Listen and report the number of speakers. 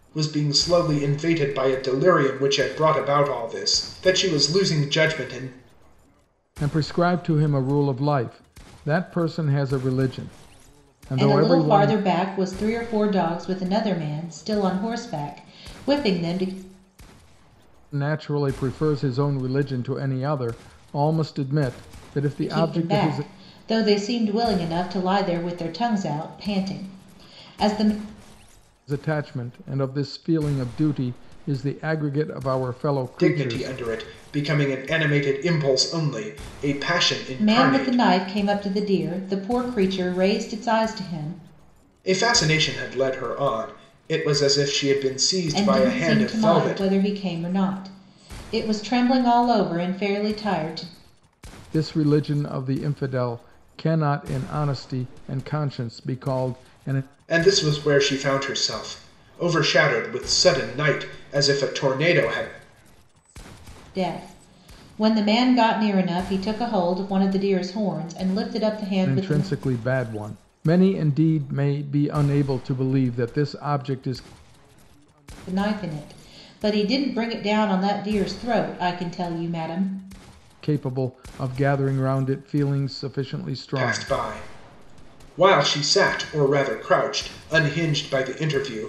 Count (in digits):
3